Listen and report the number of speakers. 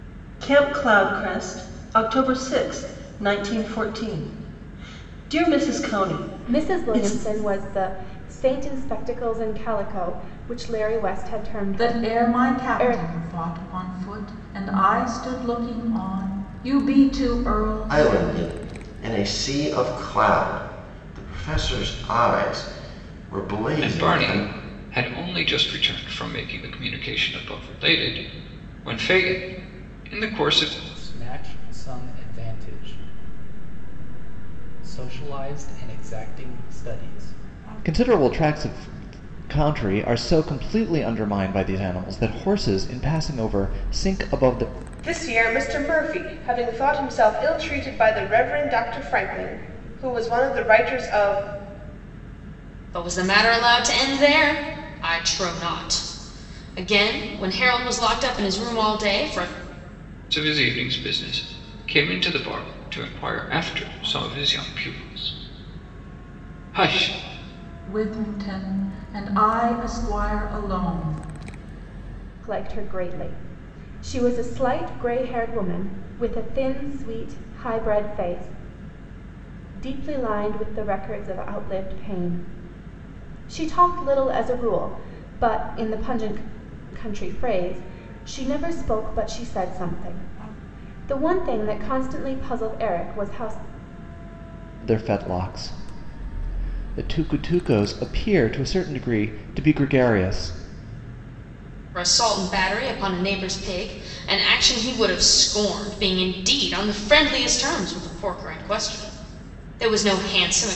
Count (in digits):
9